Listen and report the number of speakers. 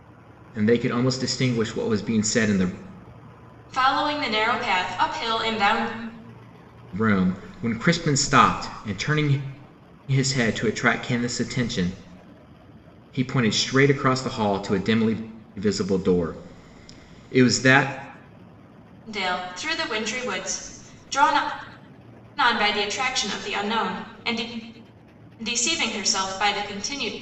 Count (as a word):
two